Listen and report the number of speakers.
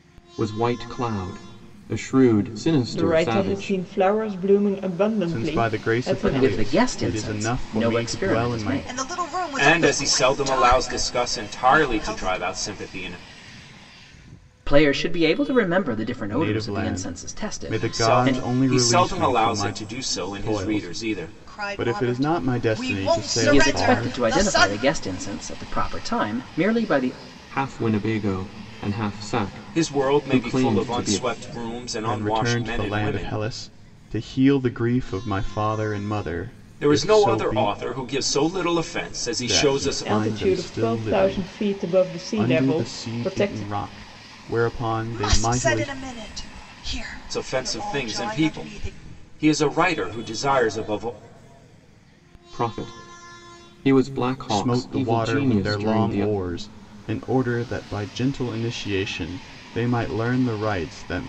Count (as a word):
six